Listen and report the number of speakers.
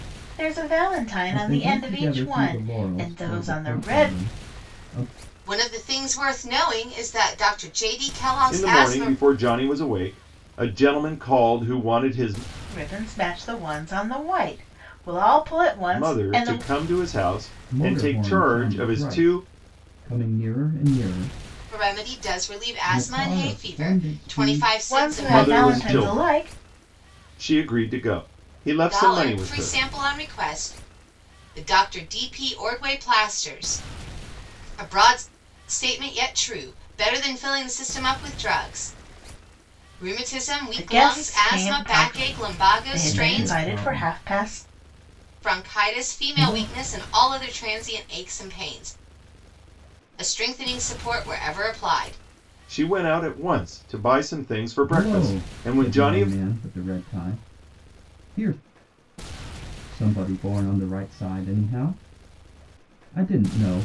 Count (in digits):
4